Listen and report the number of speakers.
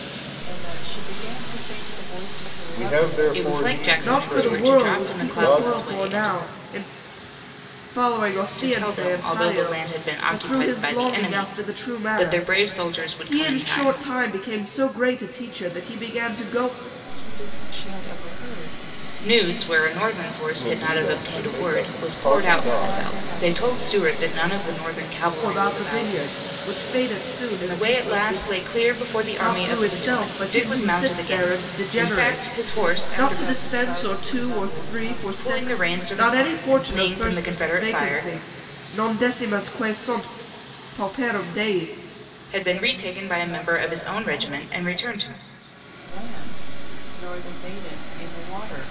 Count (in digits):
4